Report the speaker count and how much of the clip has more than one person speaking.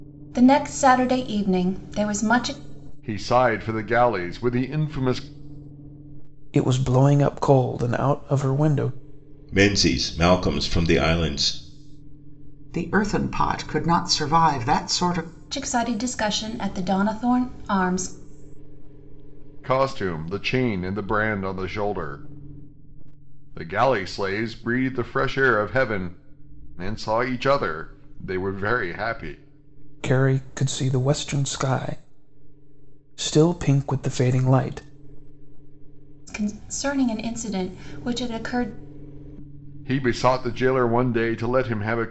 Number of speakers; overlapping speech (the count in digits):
5, no overlap